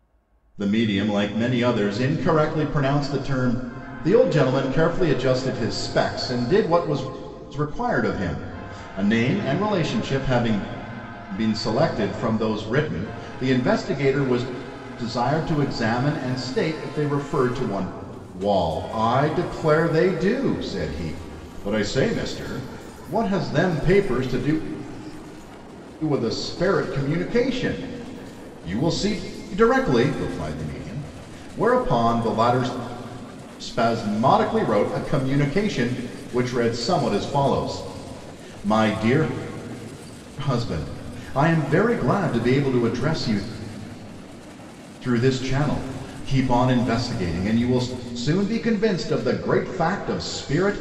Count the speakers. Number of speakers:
1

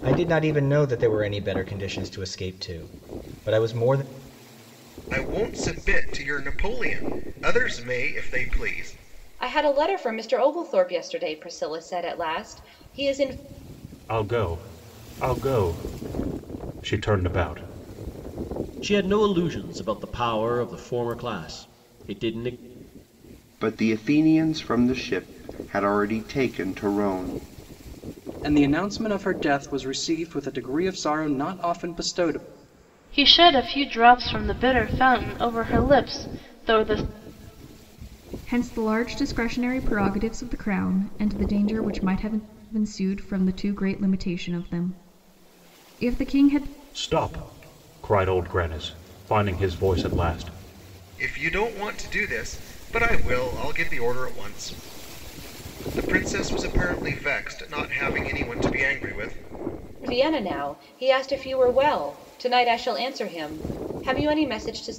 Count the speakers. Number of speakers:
9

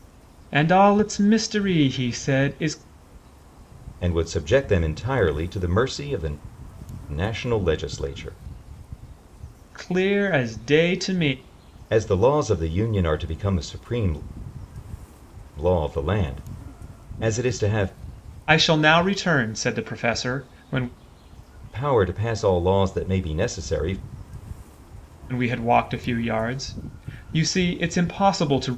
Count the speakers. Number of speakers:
2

